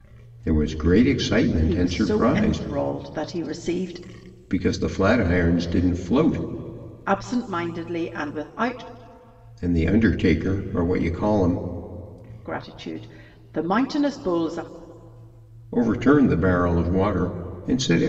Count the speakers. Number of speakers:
2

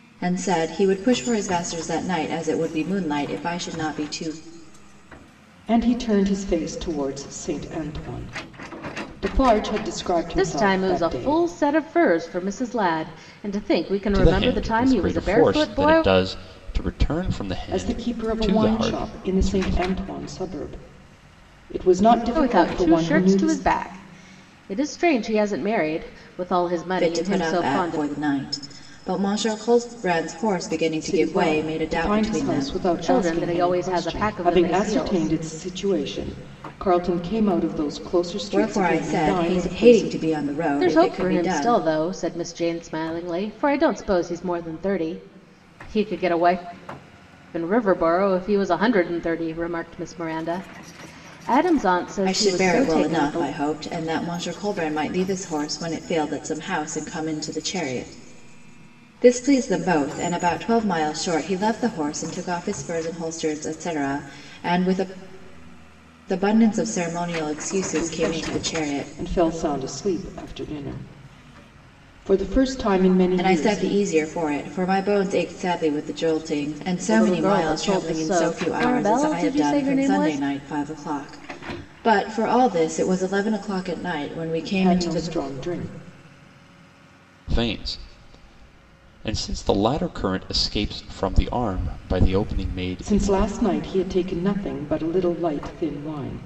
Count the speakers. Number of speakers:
4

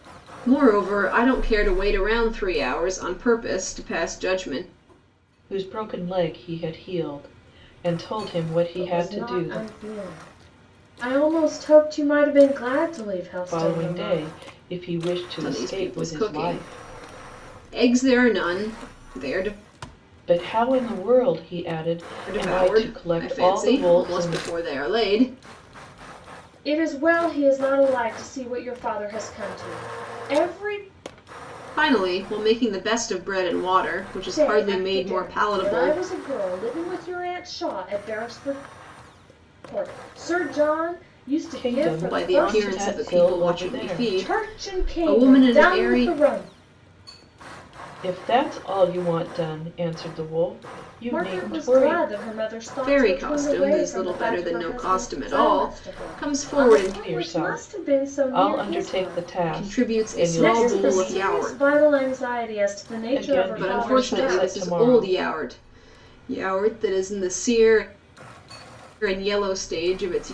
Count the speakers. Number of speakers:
3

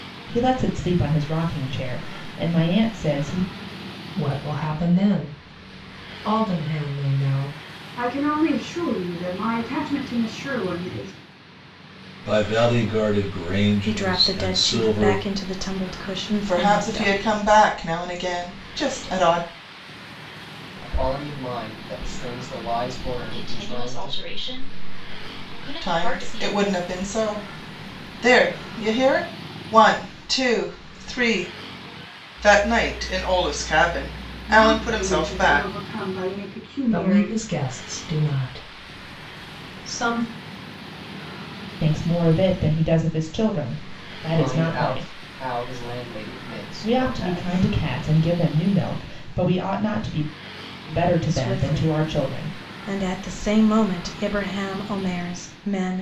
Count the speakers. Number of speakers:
8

